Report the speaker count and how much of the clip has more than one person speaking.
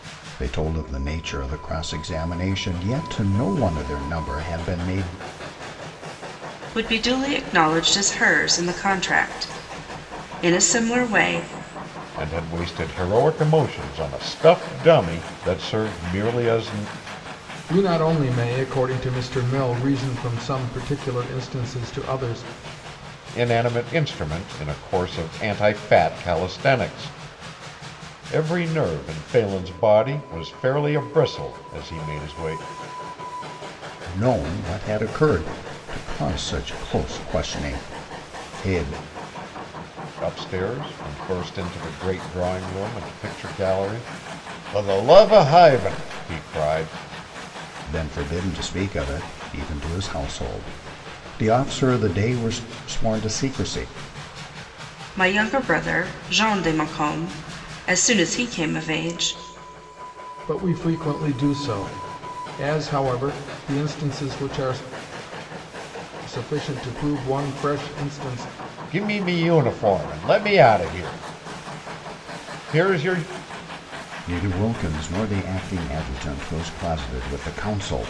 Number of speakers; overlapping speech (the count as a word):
four, no overlap